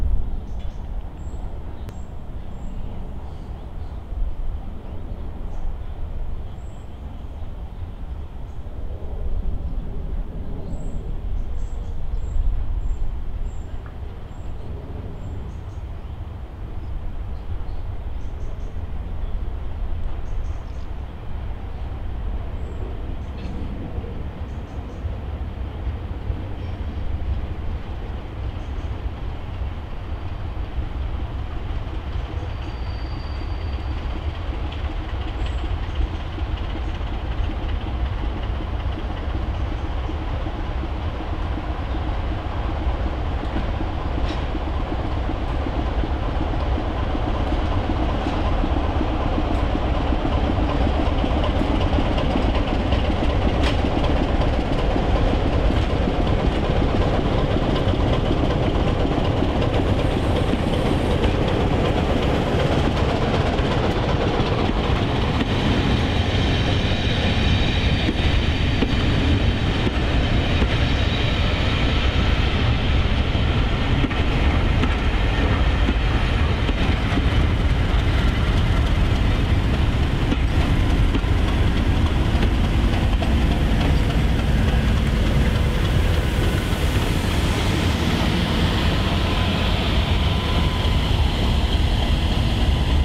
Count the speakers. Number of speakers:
zero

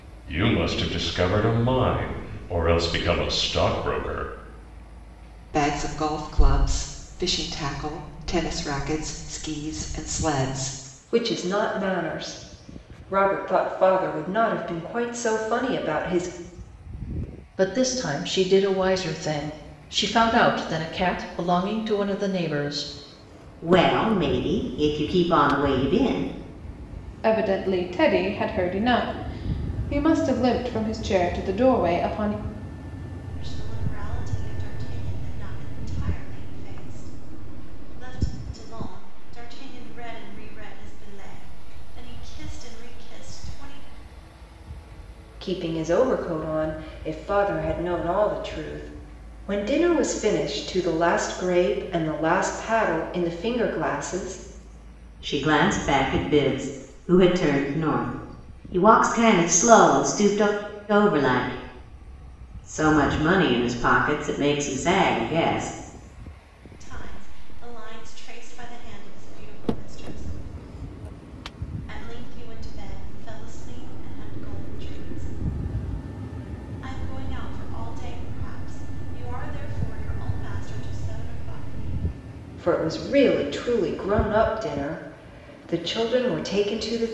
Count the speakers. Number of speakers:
seven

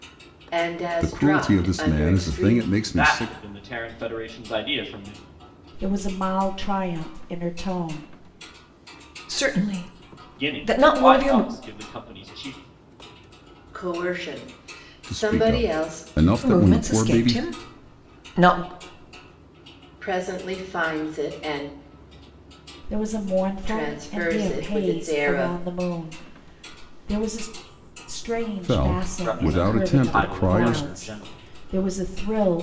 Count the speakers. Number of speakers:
five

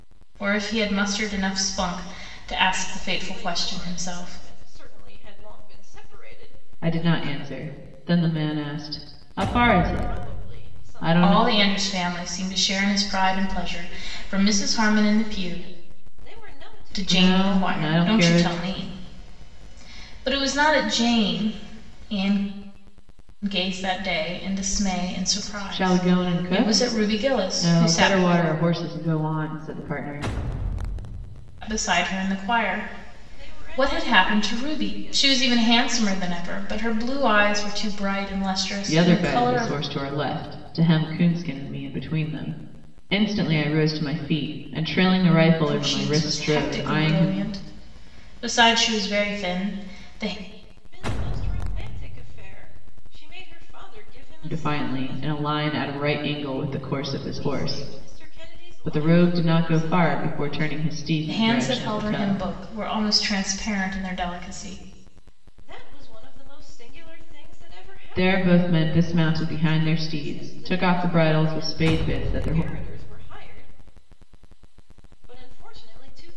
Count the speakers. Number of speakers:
three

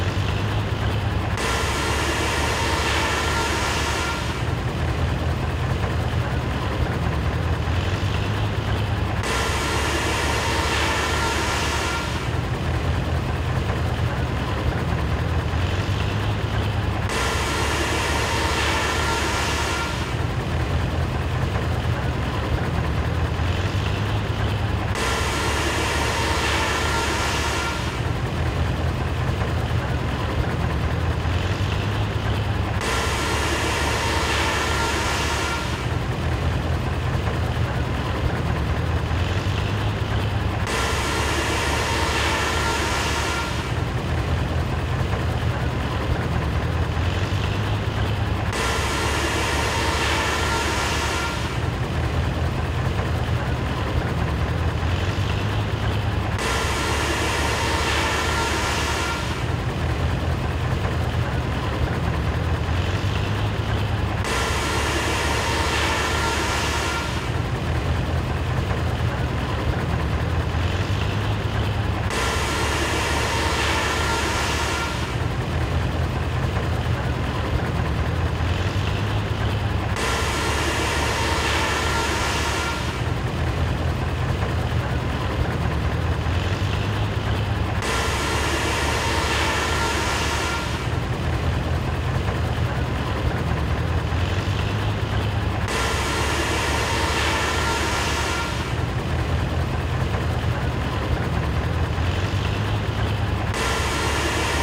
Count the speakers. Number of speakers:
zero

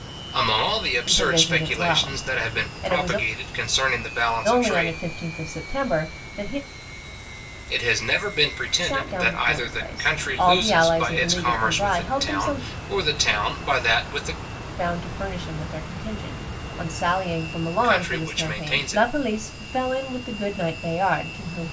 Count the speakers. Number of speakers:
two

